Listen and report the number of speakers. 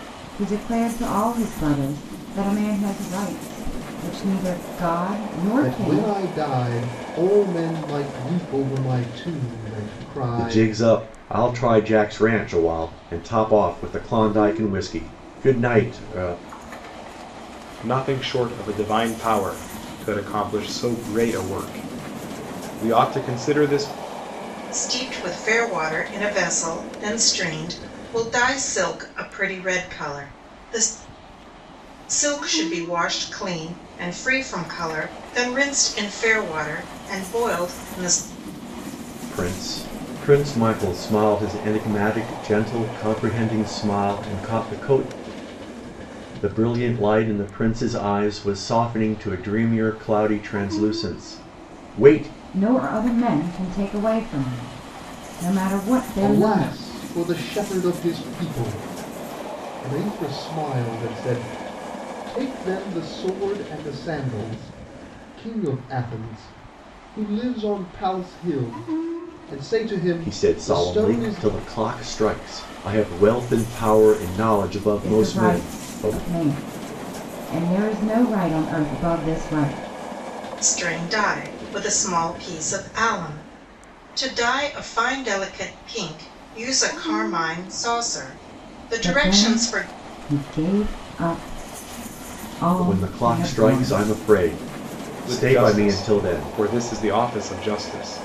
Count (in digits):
5